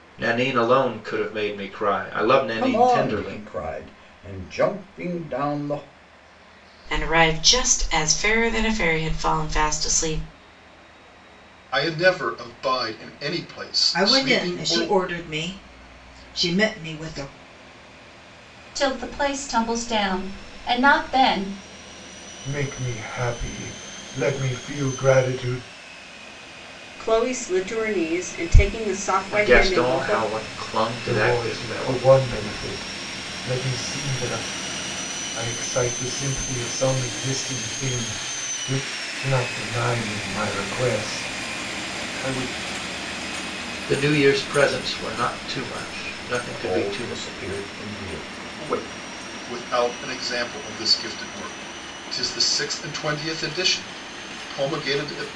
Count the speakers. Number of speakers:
8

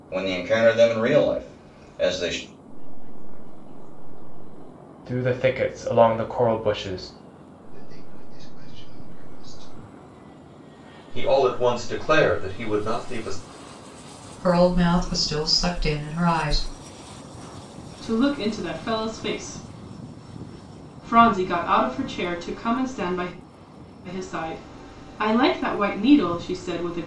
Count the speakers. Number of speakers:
7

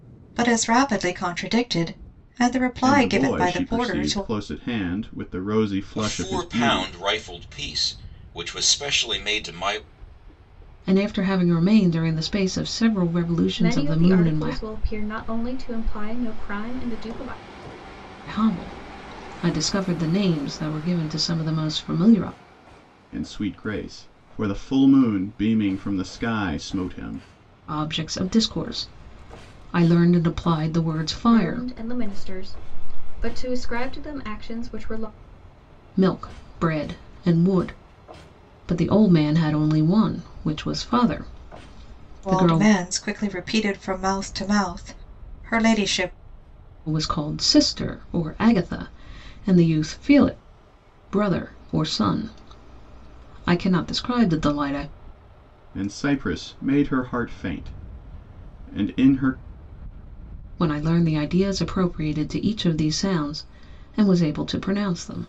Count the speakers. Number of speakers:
5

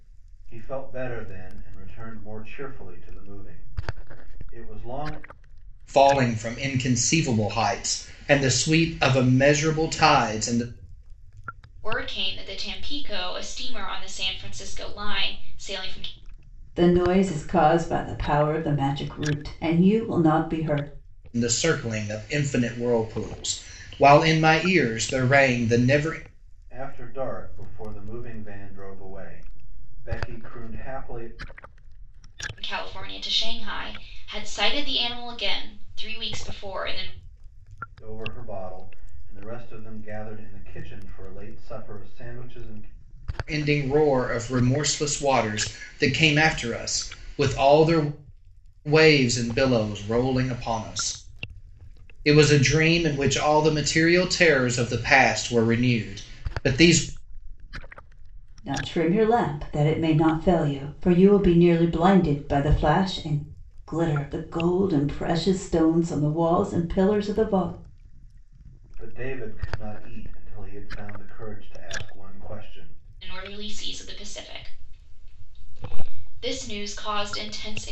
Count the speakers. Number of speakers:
4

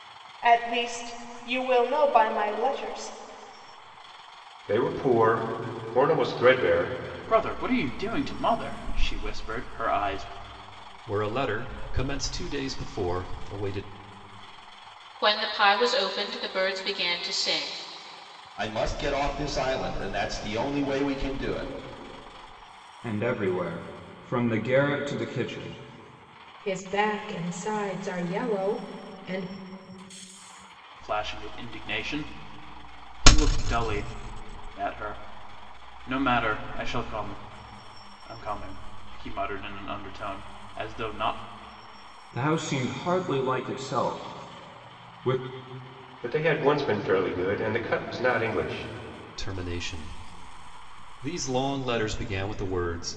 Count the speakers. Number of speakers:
8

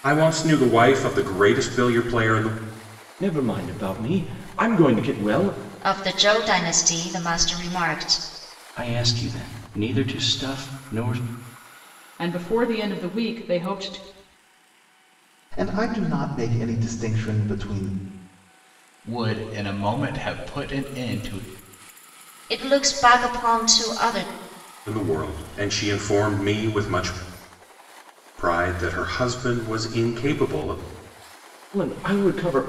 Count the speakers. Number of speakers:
7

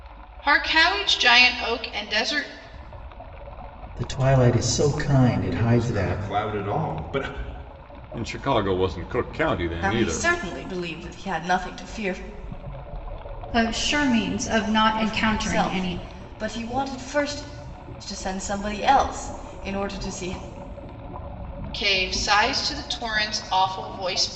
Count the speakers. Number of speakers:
6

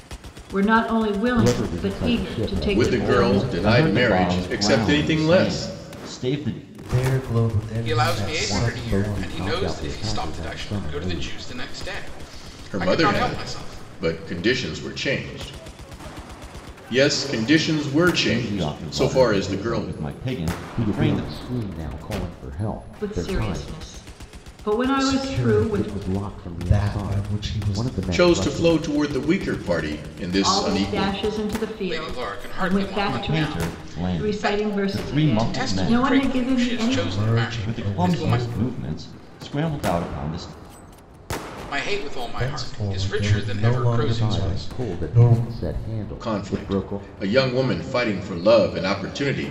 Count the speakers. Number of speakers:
6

